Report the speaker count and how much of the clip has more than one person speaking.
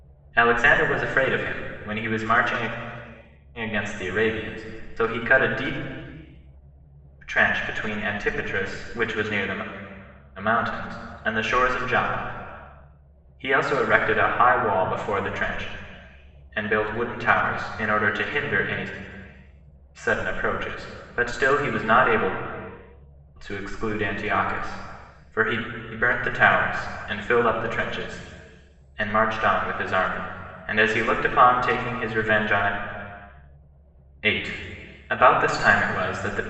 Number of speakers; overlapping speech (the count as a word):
one, no overlap